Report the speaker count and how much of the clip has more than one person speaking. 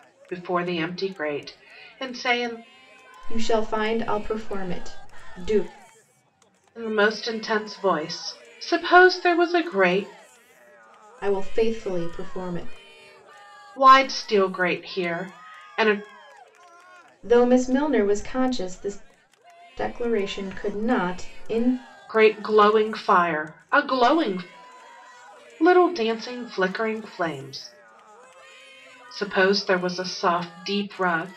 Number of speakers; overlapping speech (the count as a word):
two, no overlap